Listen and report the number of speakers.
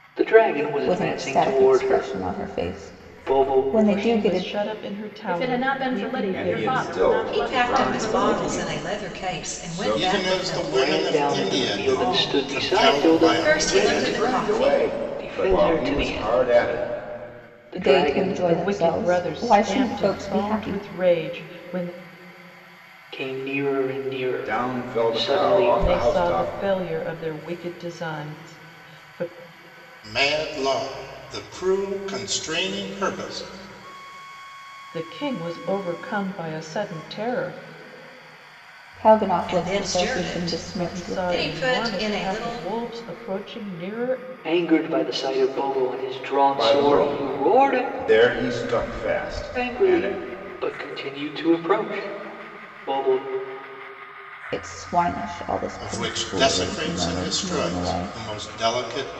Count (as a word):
seven